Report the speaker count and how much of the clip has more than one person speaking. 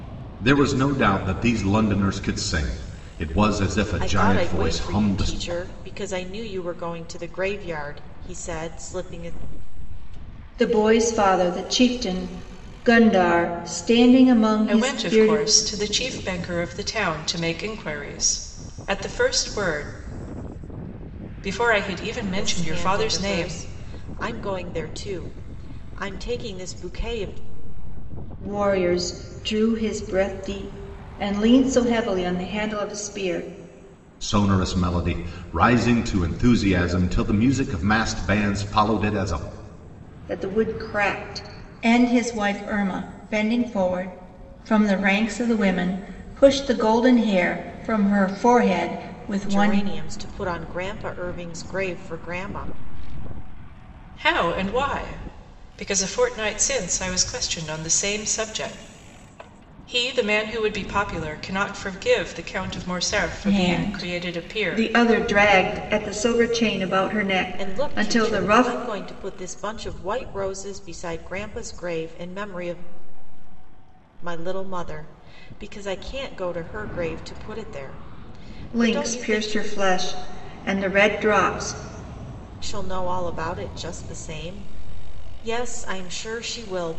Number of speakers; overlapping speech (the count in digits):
4, about 8%